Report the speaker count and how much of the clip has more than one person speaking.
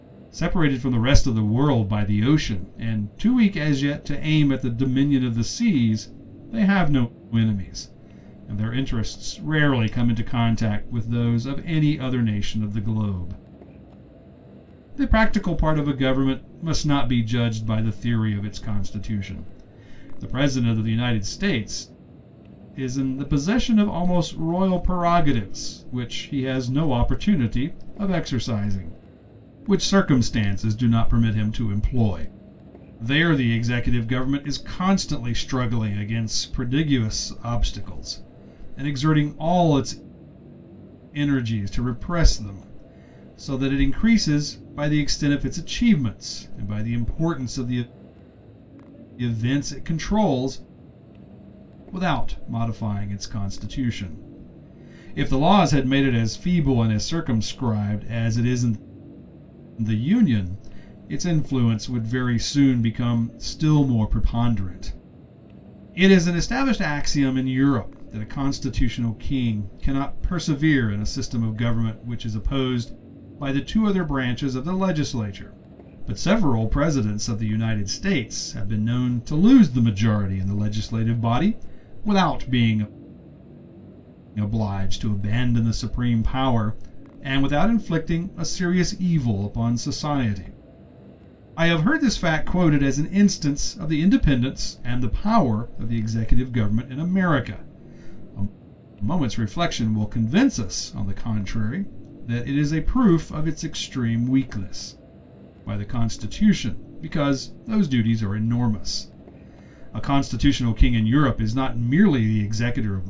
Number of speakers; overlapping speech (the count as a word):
one, no overlap